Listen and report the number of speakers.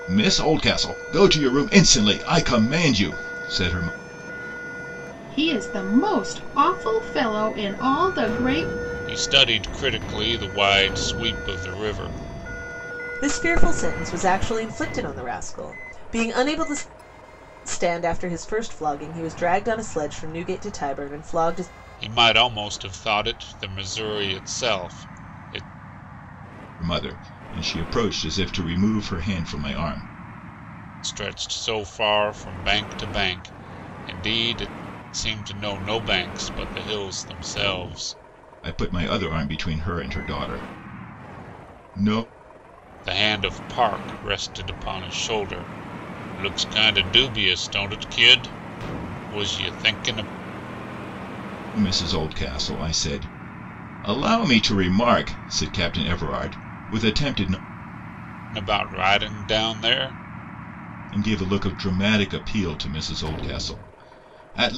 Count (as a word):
four